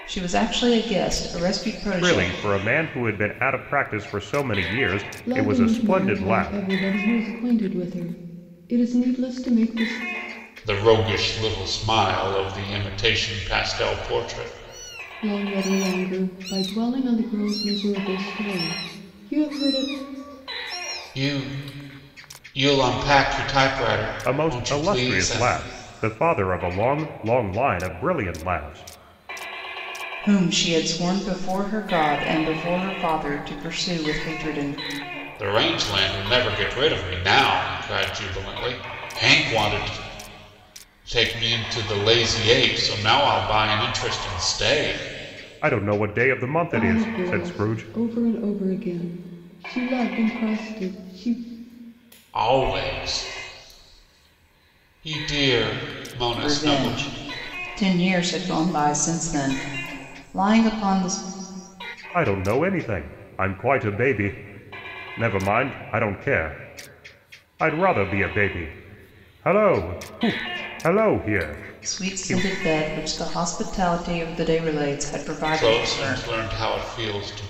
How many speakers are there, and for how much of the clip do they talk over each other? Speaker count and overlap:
4, about 8%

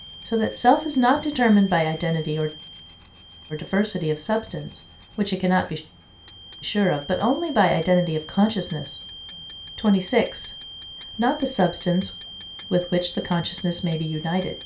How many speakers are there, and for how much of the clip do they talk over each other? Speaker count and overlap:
1, no overlap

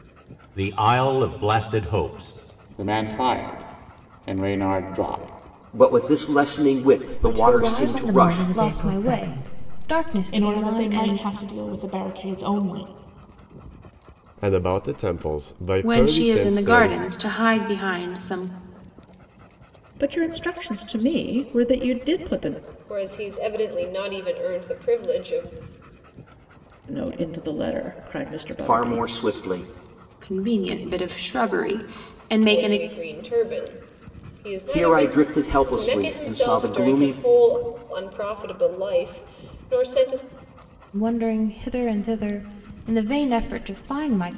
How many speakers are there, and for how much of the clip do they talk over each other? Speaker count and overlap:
10, about 17%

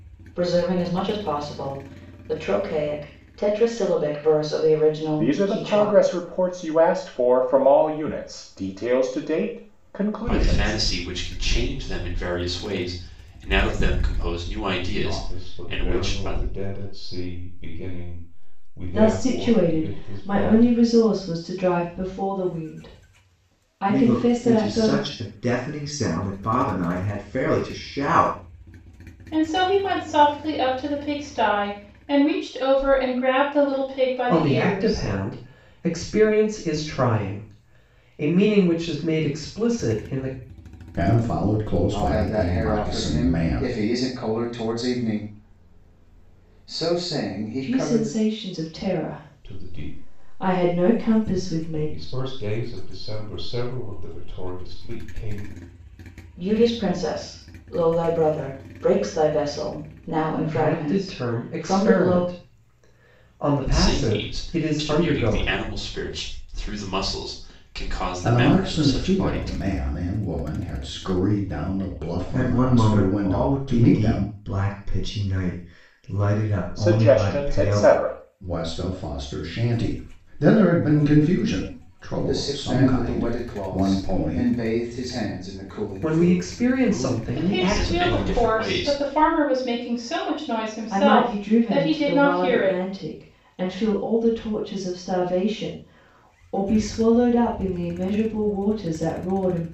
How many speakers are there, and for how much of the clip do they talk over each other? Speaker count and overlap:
10, about 28%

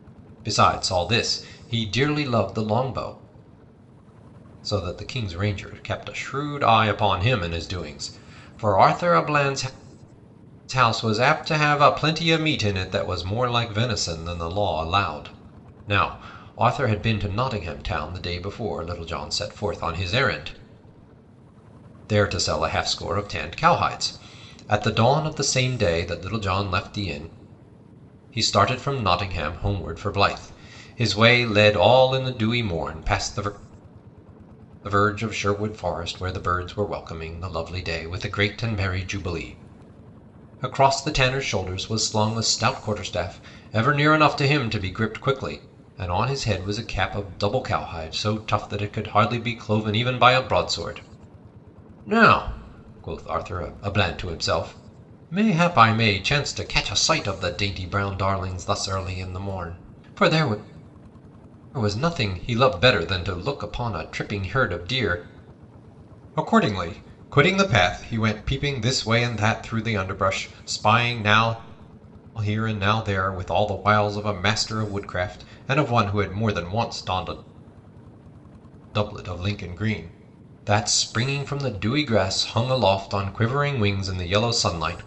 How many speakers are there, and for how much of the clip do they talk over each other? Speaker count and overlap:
1, no overlap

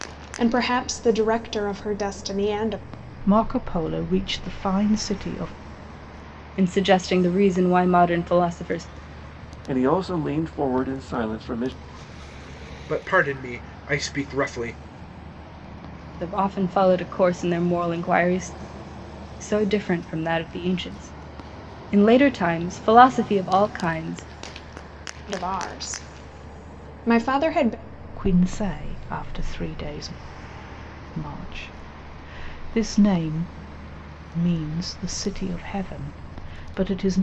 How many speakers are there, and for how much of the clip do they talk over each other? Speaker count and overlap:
5, no overlap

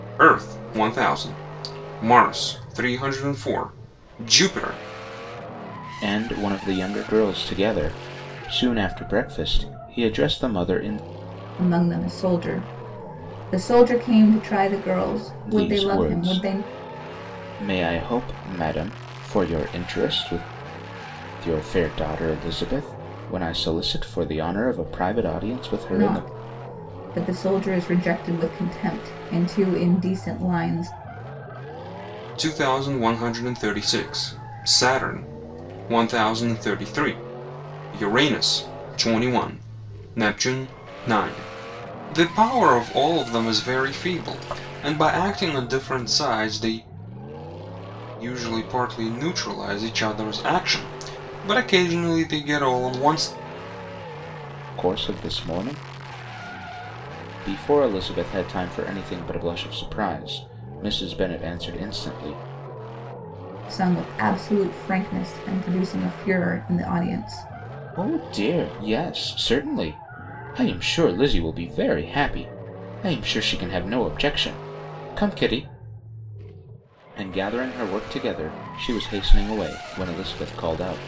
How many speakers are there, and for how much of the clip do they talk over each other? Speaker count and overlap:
3, about 2%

